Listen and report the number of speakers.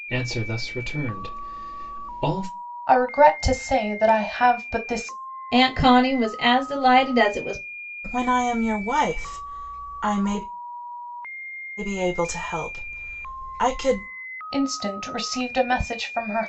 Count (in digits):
4